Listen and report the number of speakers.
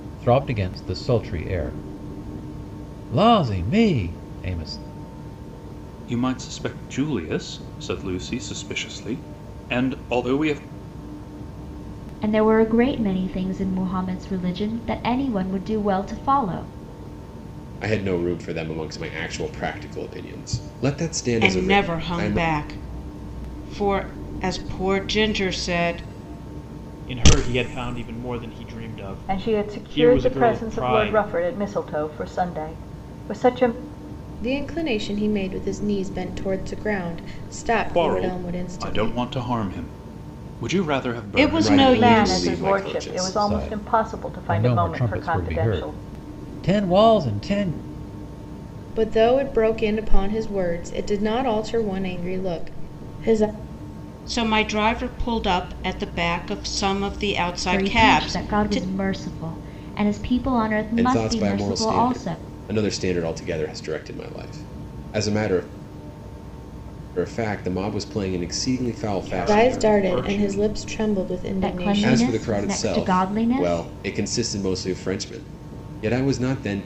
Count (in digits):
8